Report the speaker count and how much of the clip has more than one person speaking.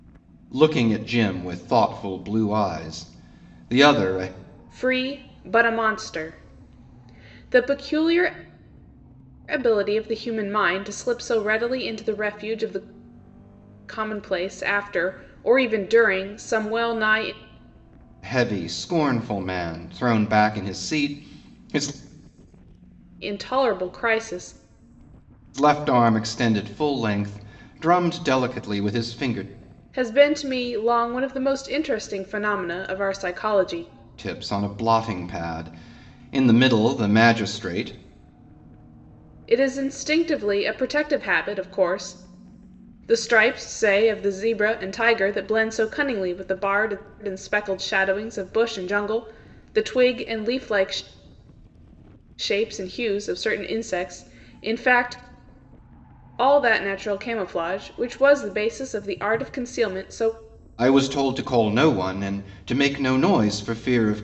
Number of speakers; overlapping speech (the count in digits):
2, no overlap